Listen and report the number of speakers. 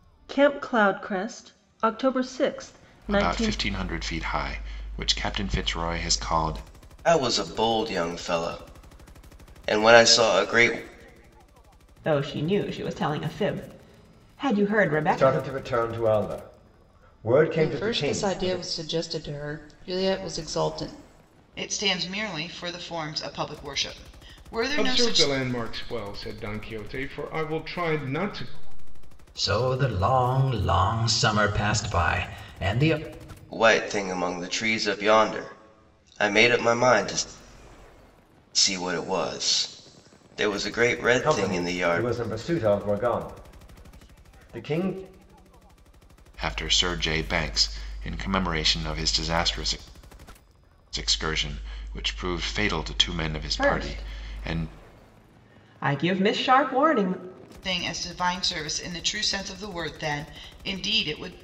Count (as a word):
nine